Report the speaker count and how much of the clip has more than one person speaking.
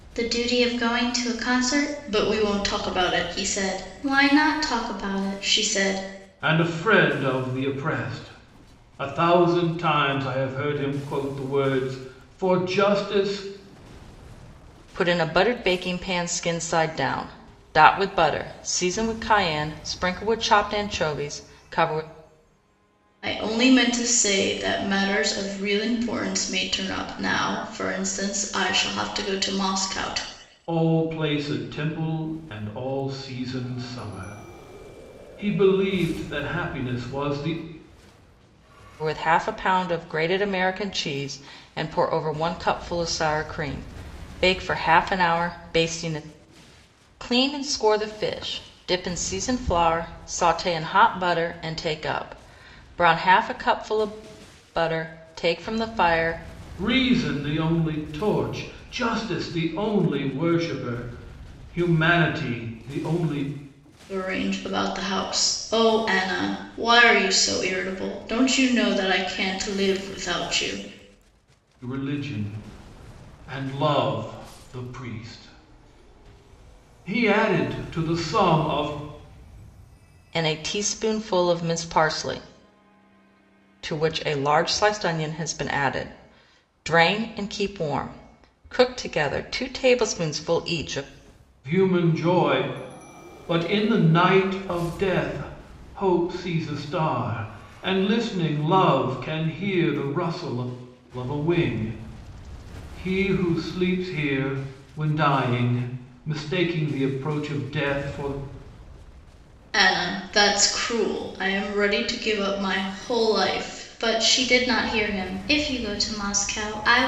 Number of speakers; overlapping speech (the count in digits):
3, no overlap